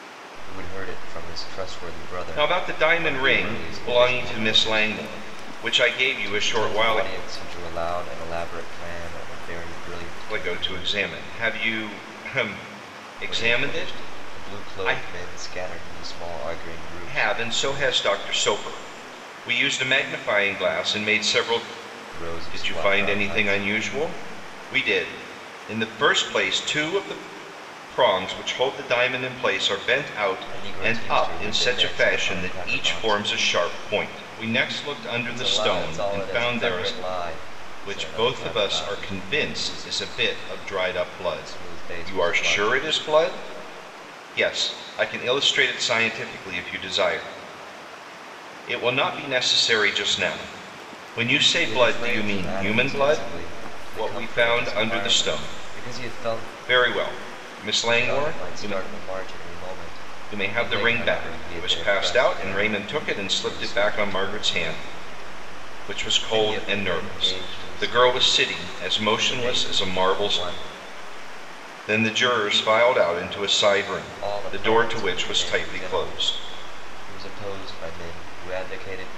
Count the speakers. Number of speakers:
2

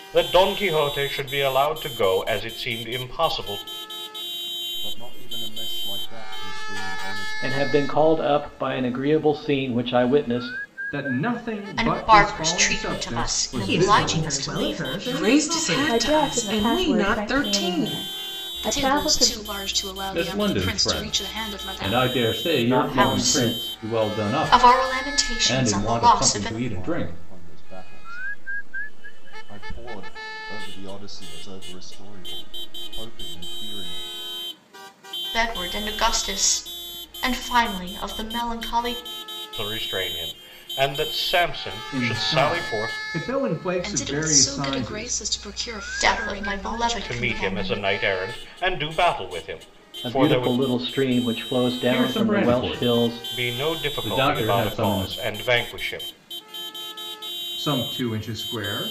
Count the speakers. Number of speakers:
10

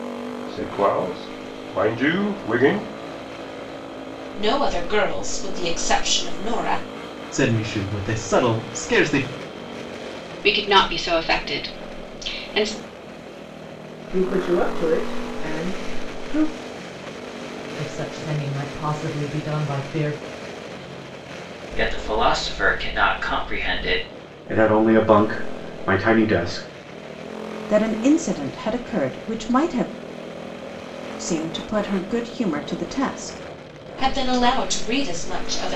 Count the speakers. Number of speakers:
9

